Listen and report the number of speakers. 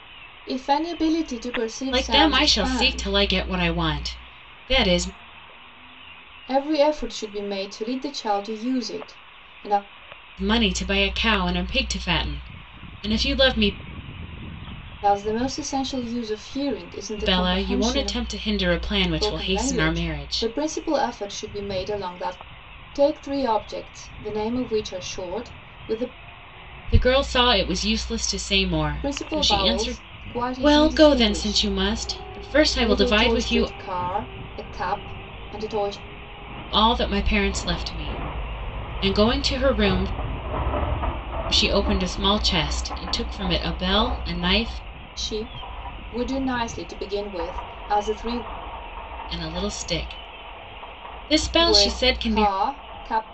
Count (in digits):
2